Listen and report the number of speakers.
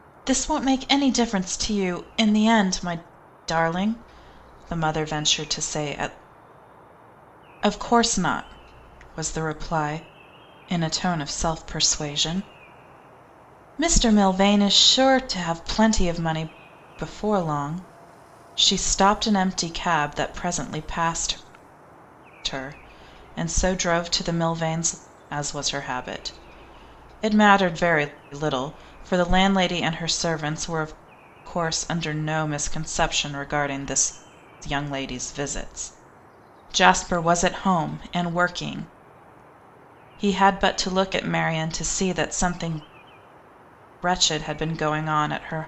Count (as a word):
one